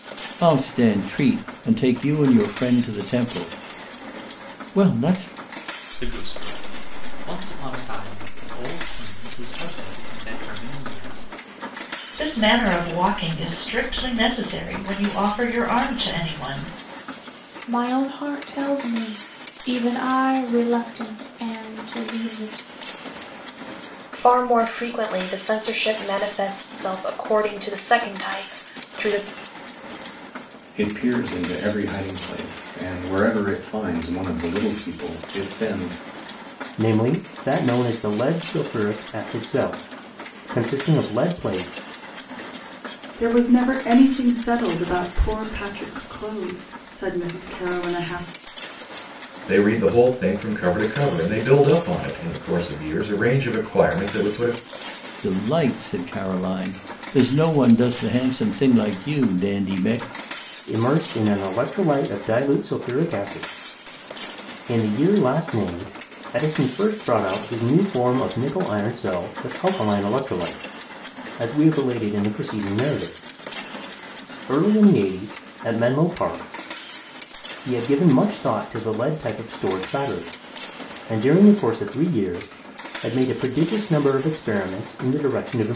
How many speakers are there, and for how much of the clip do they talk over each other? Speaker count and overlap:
nine, no overlap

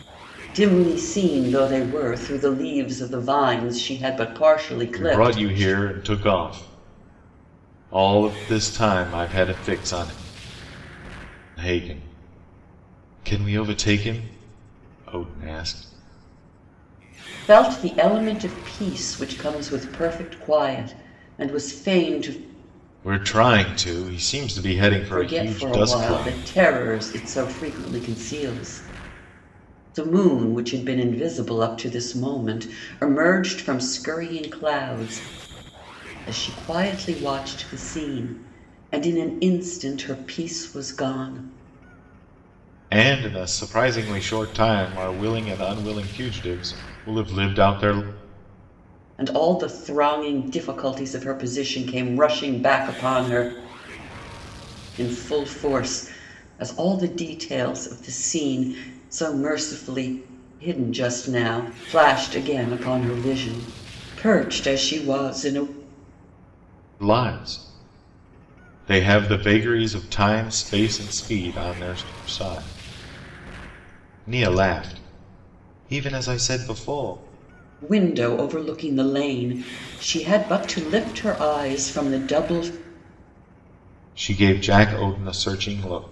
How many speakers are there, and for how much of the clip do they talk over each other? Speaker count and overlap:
two, about 3%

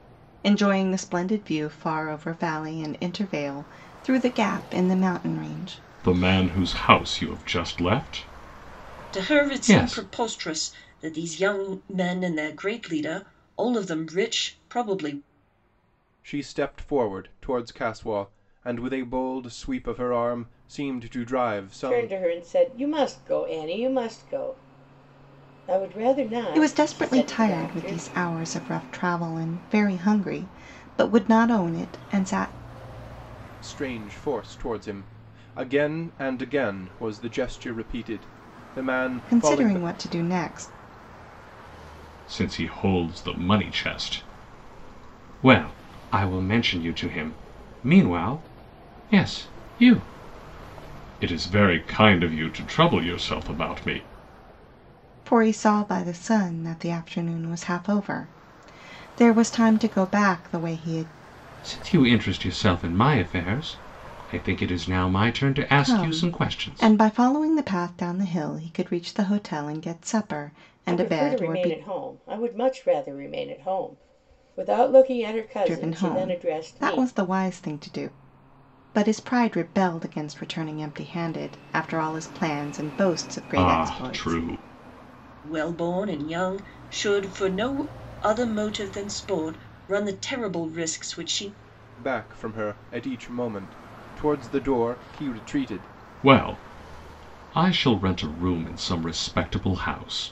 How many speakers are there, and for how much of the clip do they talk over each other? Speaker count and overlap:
five, about 9%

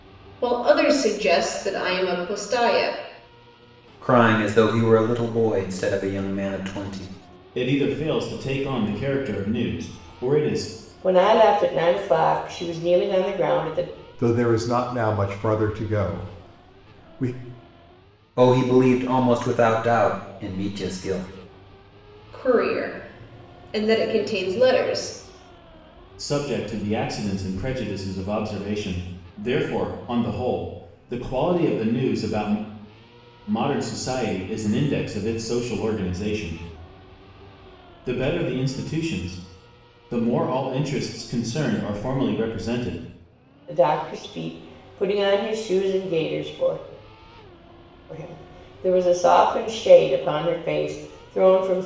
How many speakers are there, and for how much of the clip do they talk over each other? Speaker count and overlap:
five, no overlap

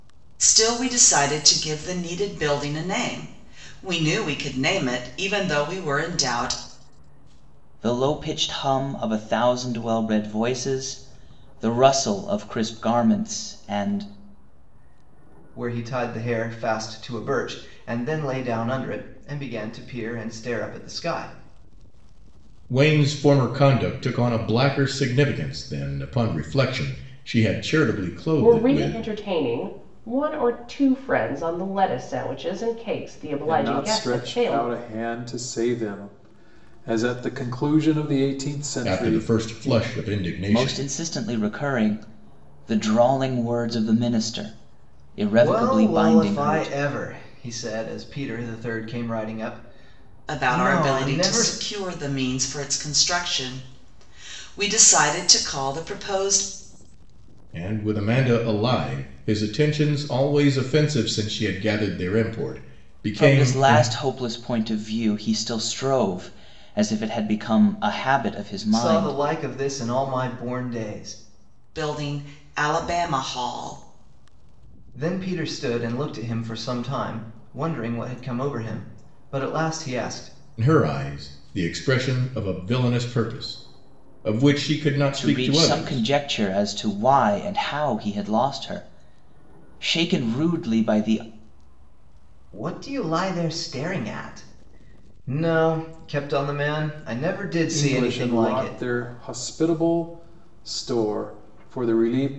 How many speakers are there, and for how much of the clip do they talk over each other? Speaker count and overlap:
six, about 9%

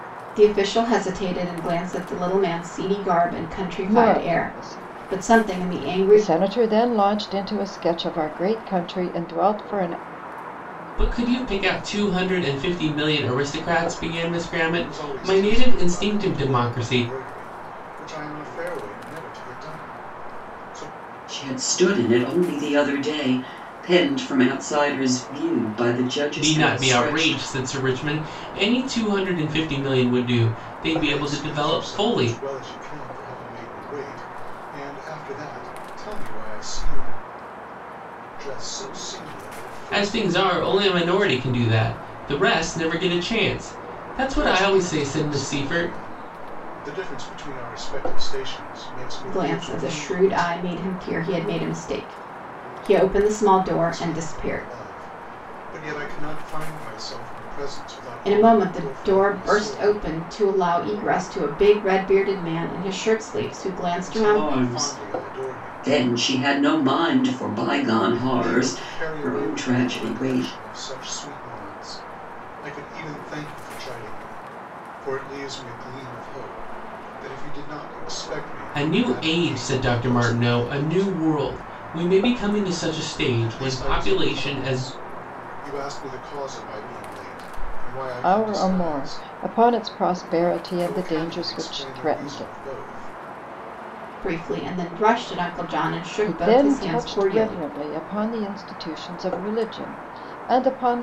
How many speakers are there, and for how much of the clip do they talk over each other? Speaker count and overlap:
five, about 27%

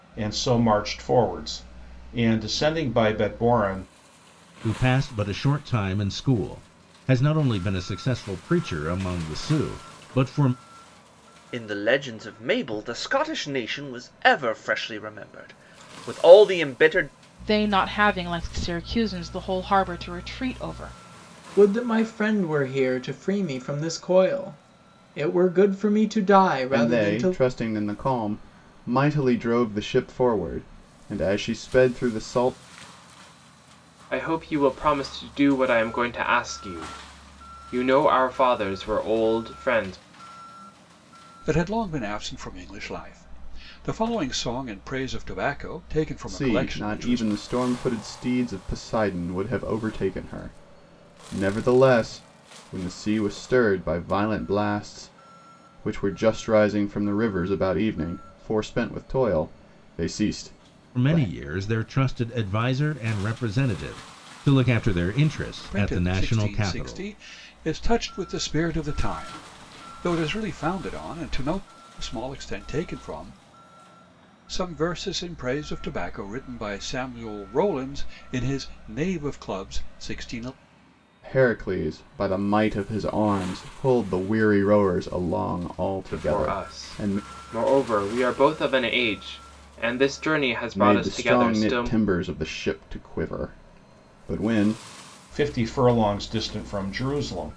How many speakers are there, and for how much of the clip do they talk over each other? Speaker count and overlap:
eight, about 6%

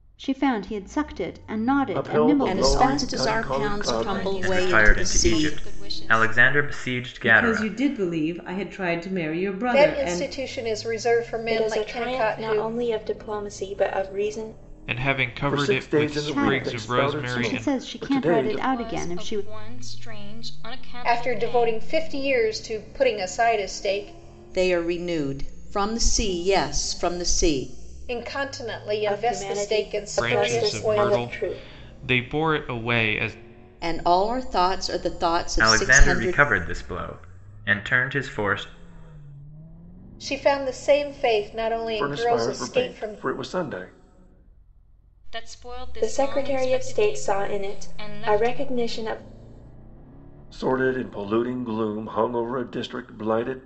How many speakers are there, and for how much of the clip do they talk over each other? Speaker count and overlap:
nine, about 36%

